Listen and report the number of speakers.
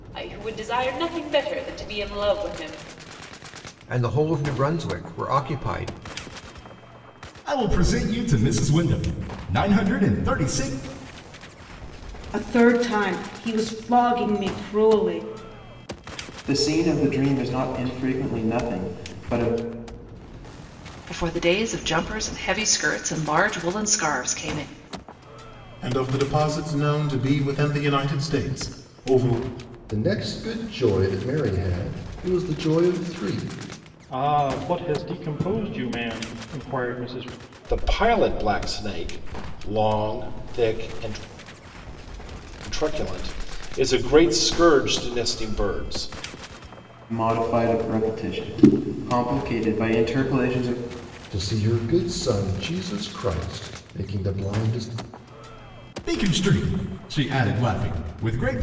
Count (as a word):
ten